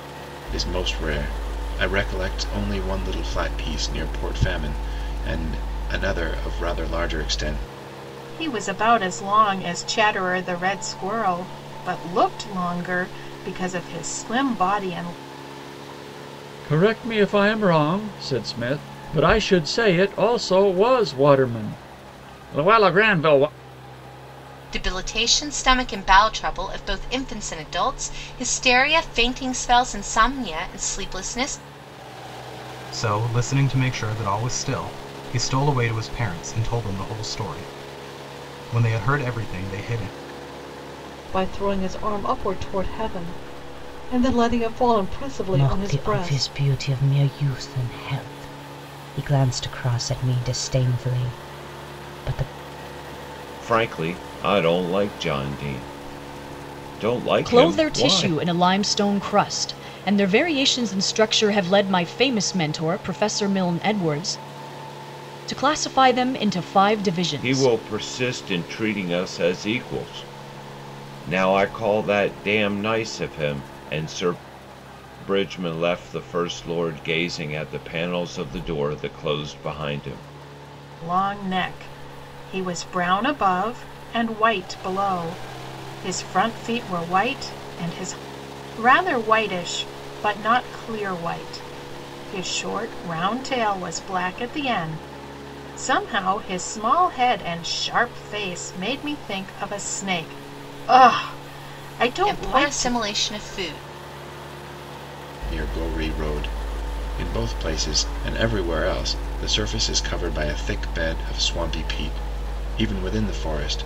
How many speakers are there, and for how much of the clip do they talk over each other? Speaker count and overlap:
nine, about 3%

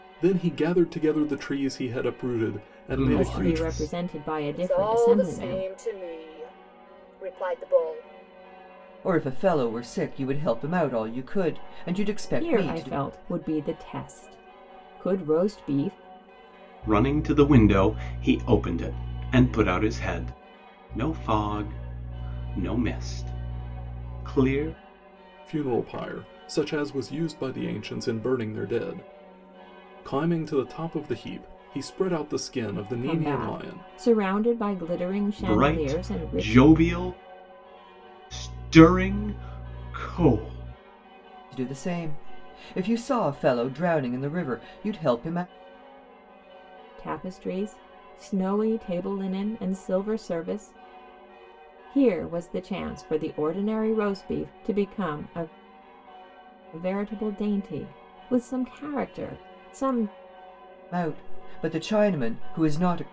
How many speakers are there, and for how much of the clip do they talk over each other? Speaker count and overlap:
five, about 8%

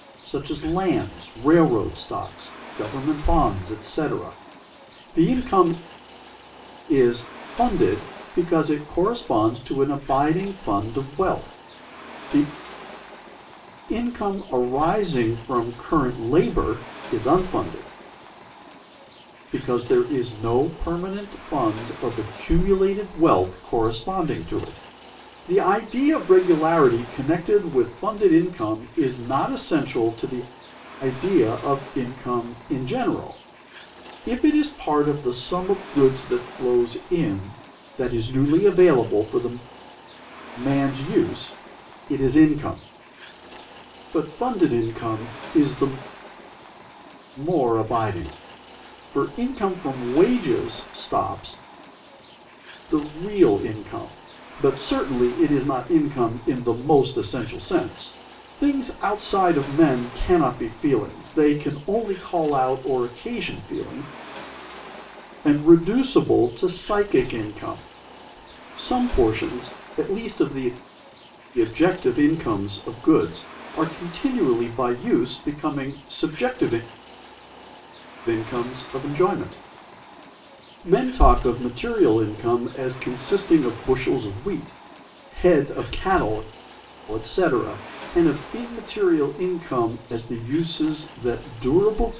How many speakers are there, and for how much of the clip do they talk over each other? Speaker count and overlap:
one, no overlap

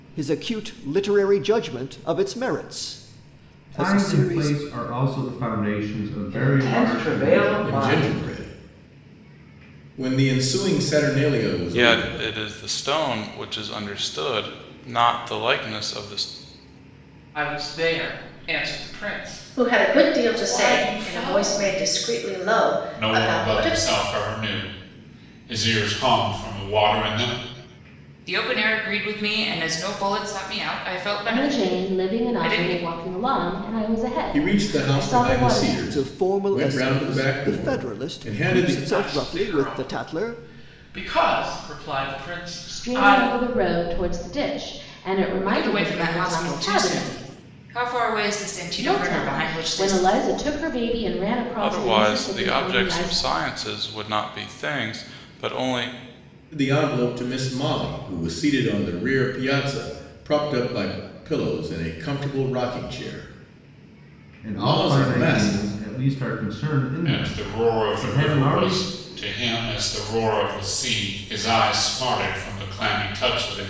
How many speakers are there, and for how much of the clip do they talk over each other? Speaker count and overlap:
ten, about 30%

